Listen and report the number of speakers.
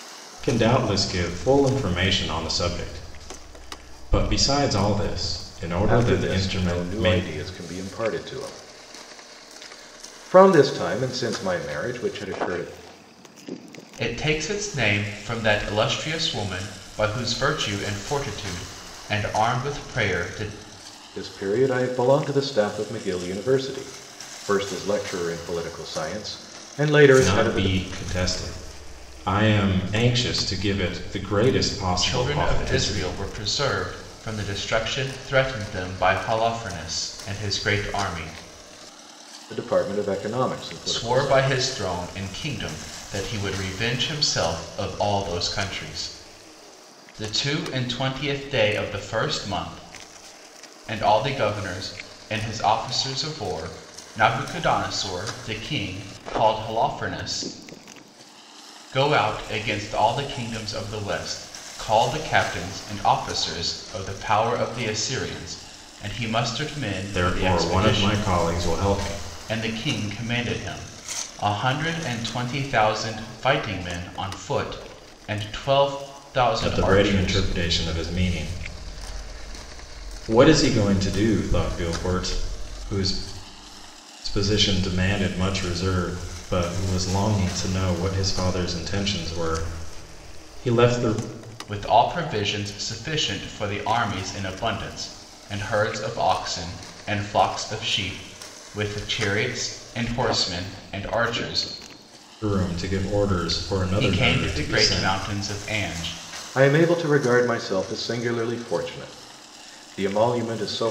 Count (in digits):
3